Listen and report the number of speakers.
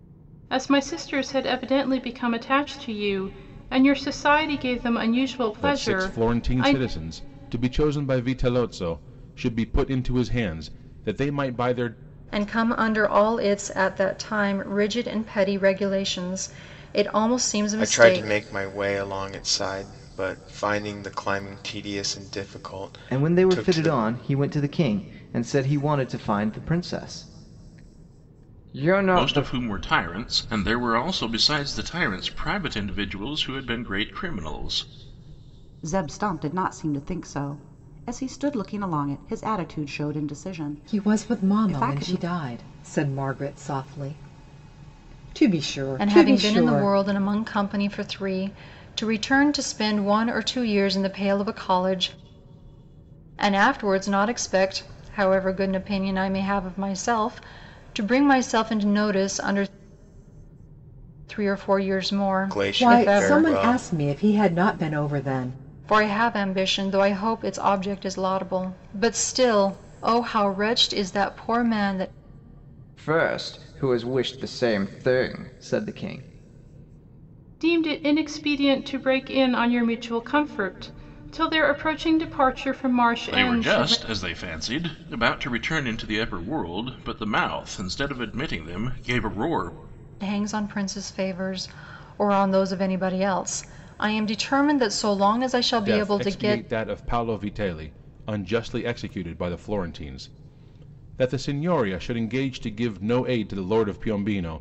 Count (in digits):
8